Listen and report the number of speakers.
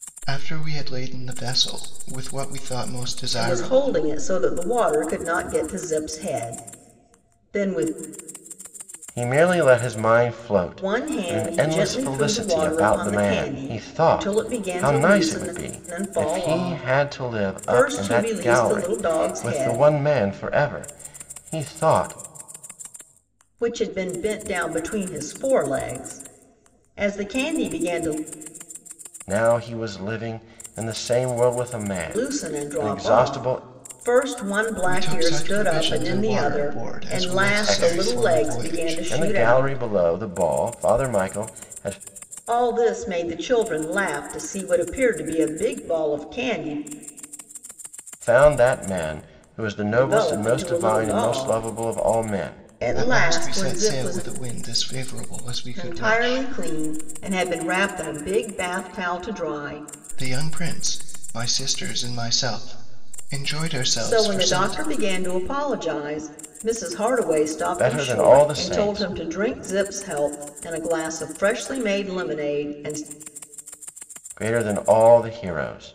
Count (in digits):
3